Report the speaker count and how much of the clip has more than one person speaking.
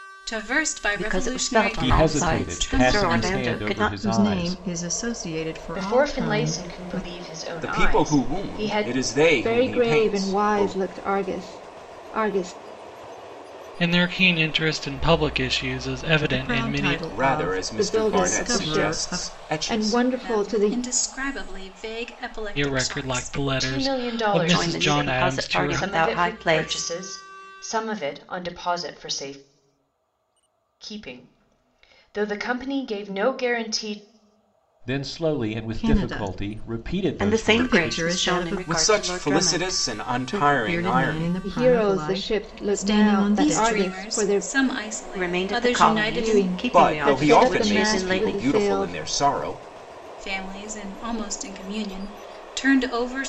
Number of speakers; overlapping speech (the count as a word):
eight, about 54%